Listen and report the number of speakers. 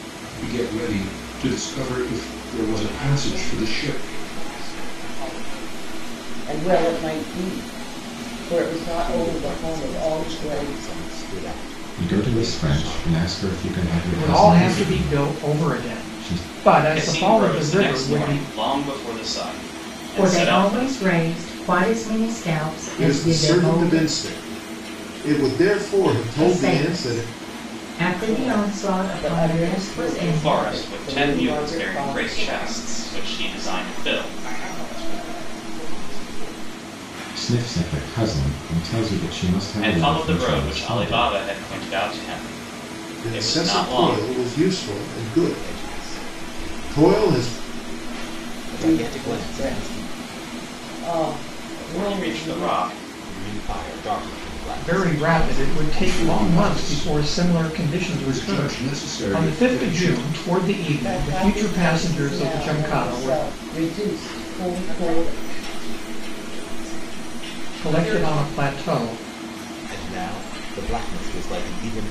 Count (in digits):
9